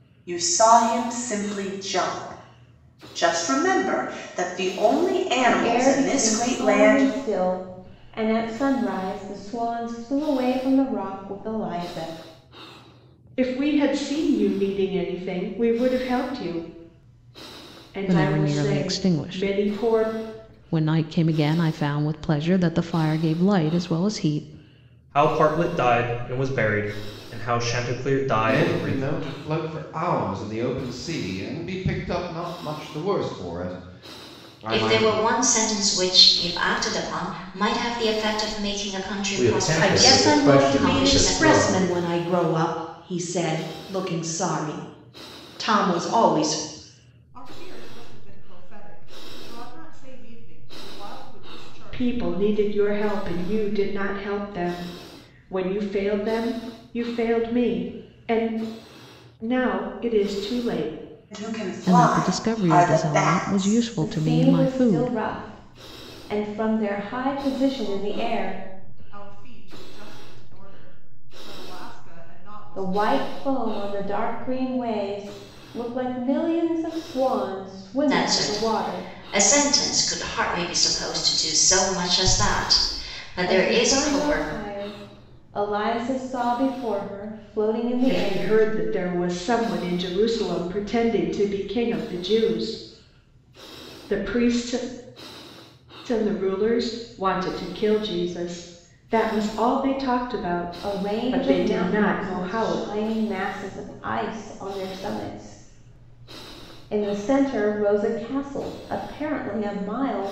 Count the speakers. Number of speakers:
10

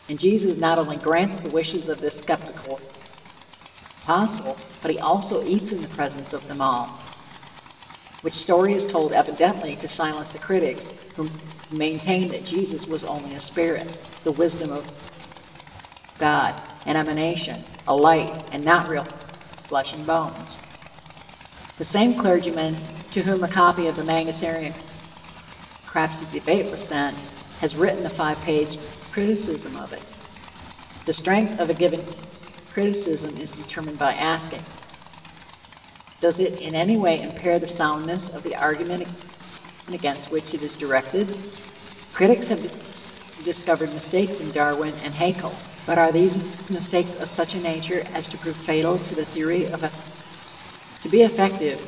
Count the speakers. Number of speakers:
1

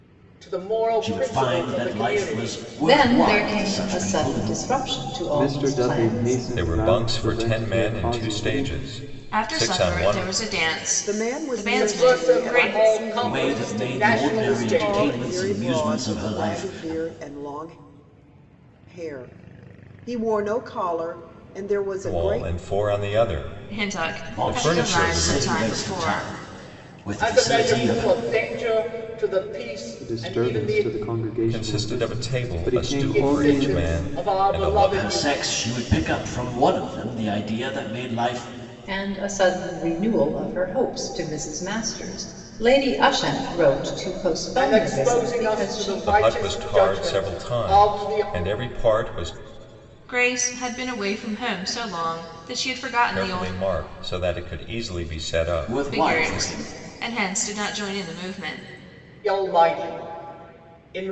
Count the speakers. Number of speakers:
7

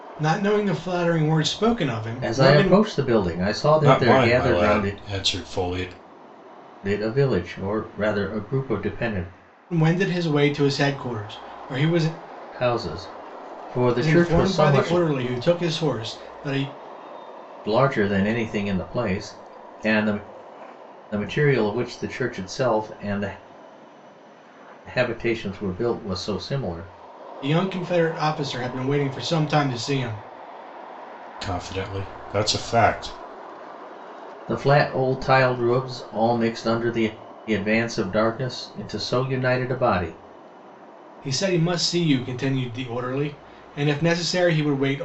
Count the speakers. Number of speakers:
3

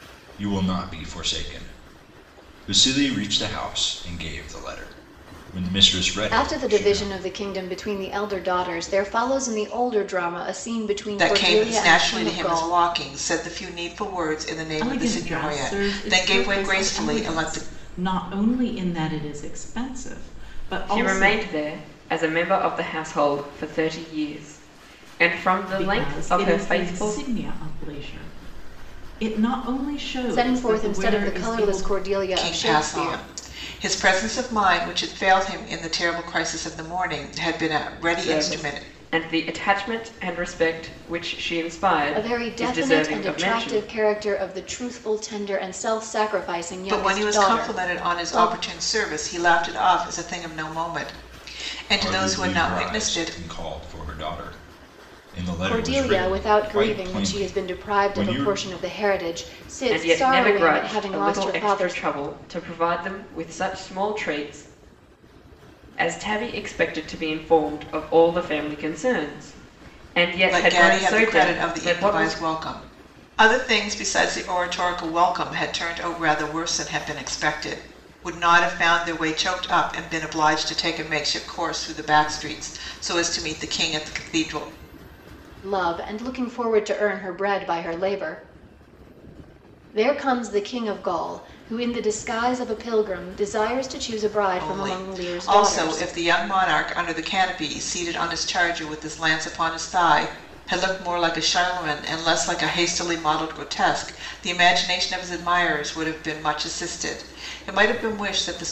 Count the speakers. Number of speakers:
5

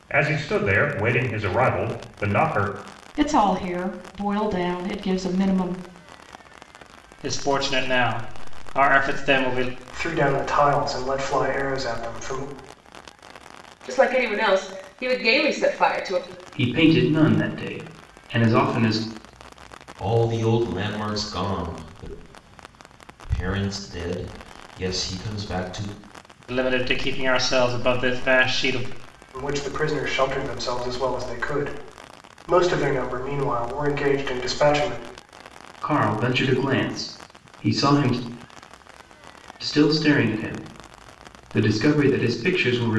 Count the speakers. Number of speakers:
7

